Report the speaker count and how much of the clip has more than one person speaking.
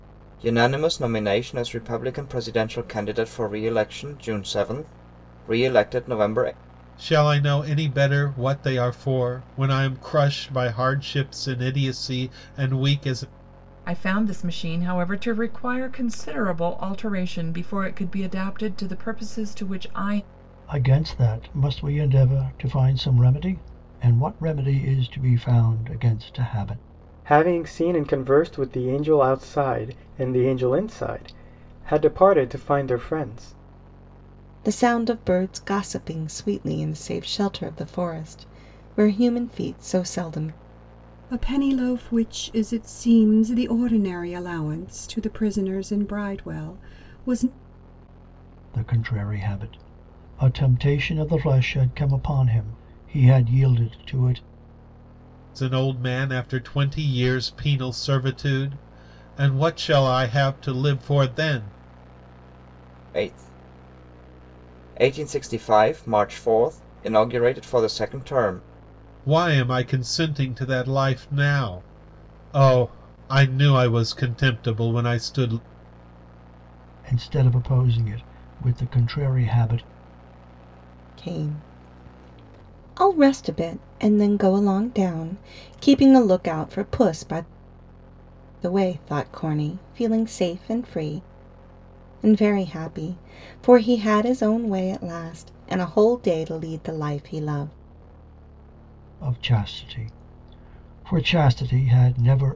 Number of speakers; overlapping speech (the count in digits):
7, no overlap